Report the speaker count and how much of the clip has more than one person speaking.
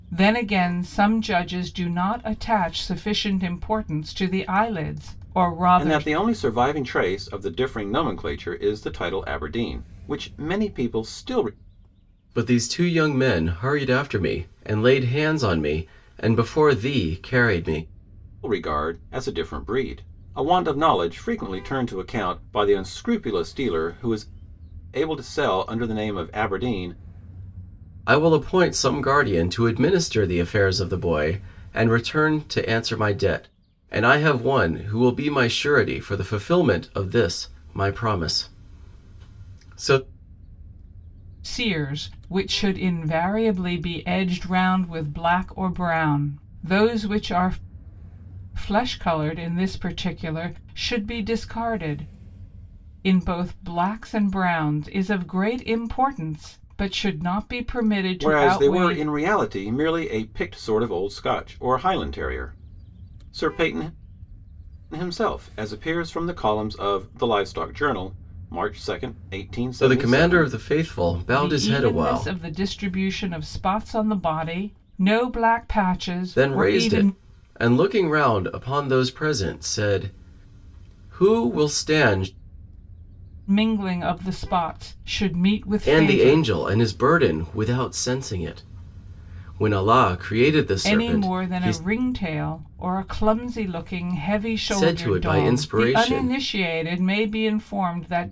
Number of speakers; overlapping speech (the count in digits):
3, about 7%